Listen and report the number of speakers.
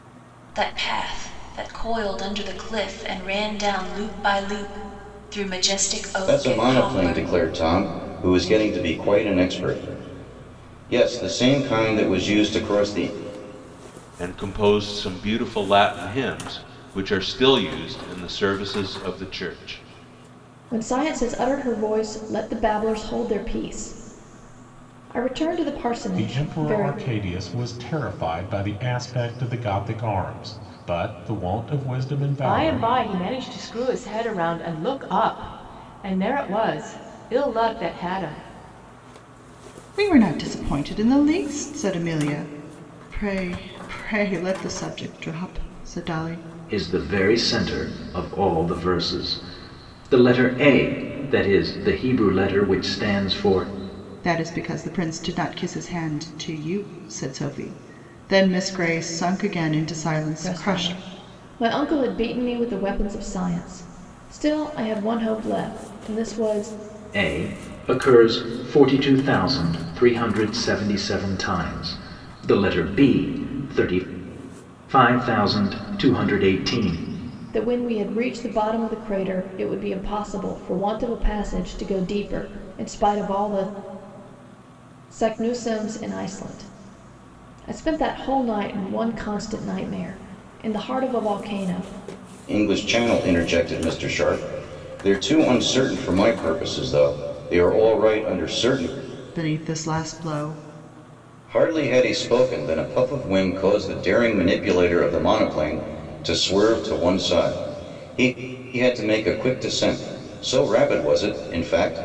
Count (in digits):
8